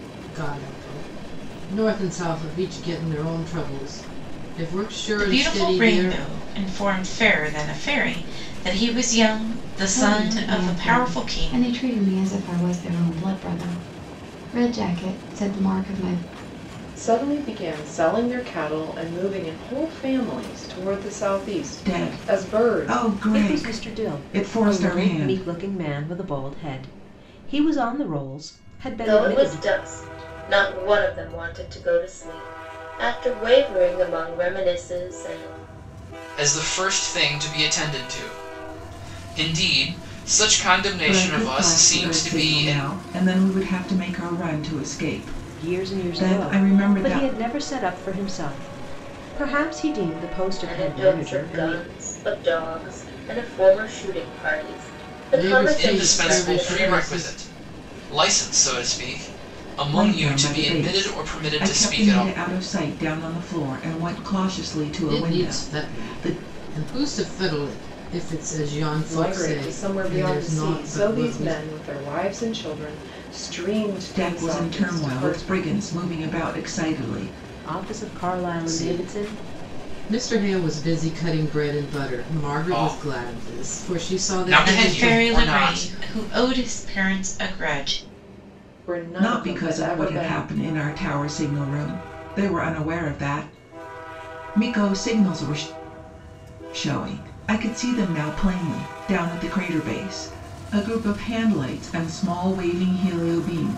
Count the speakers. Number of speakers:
eight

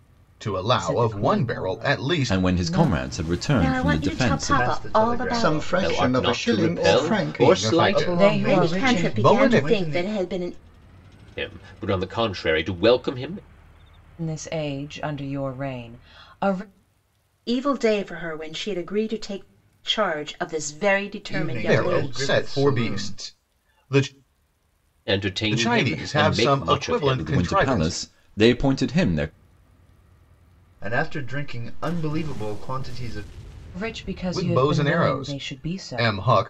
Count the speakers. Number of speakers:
seven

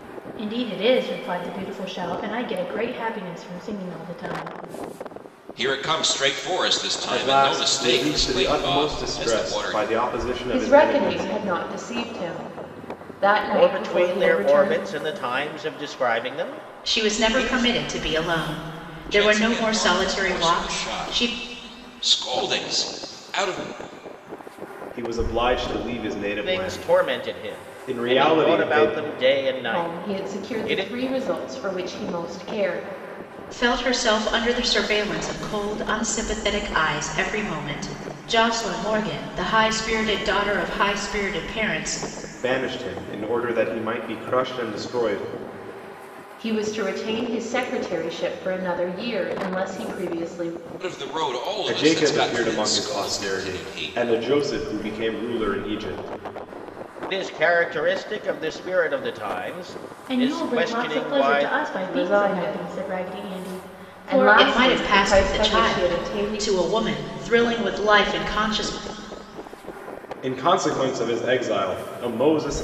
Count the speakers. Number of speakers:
six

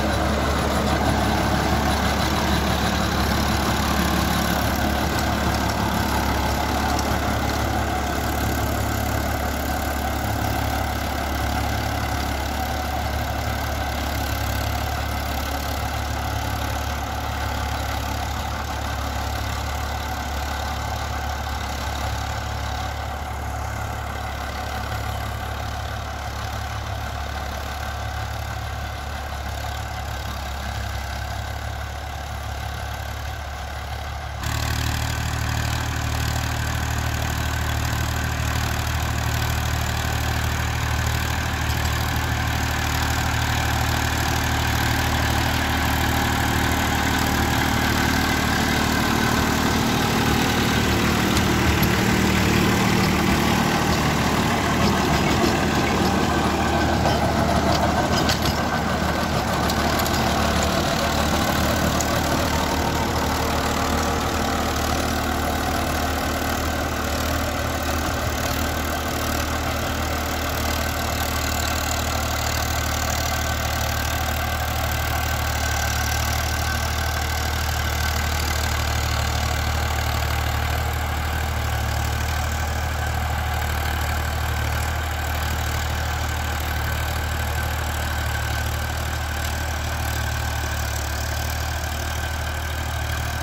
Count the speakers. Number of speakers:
zero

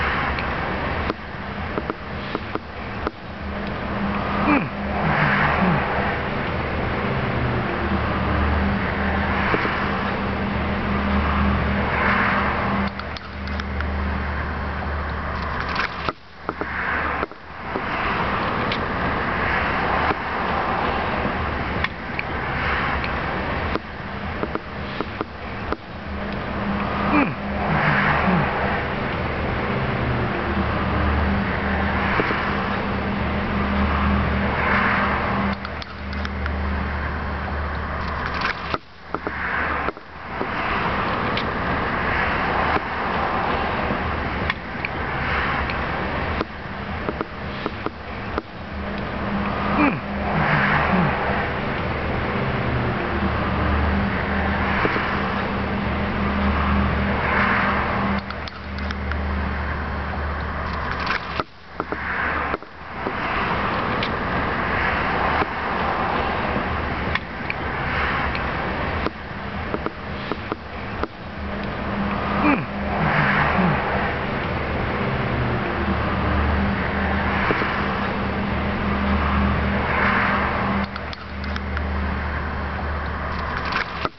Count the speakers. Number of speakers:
zero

